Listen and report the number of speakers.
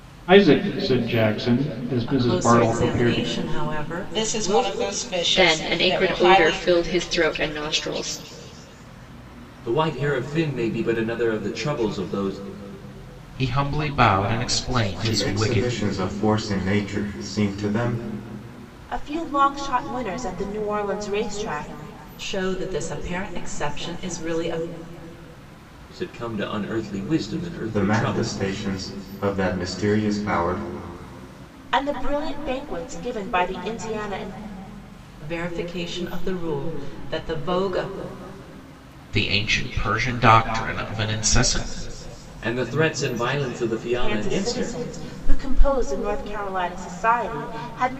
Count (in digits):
8